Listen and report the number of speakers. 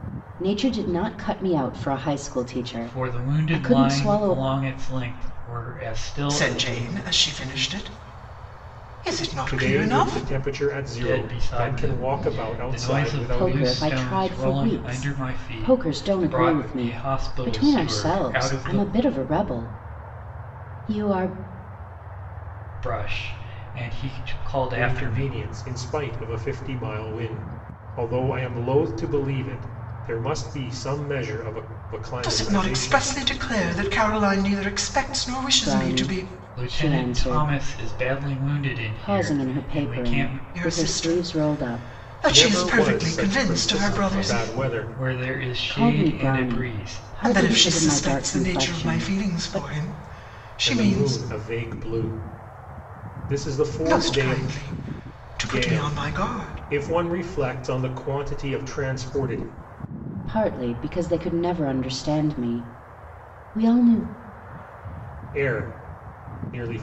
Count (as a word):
four